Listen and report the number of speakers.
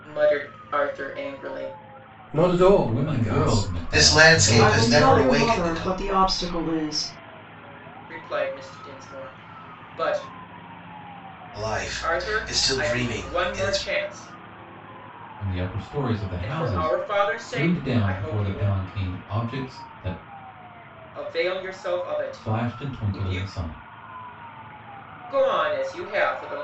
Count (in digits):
5